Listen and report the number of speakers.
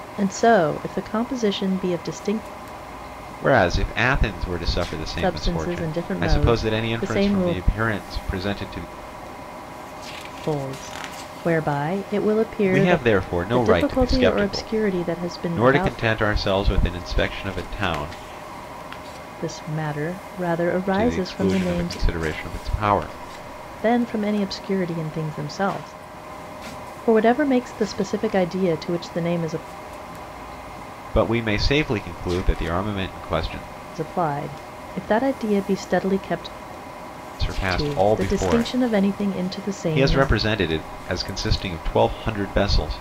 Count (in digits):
2